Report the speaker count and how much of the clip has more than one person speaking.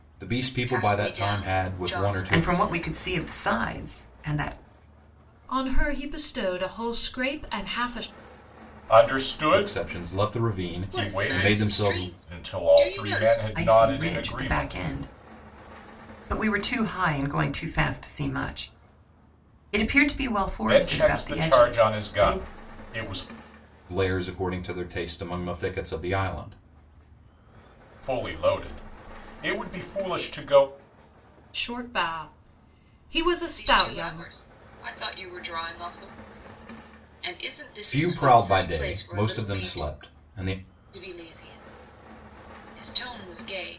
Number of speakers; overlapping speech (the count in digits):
5, about 27%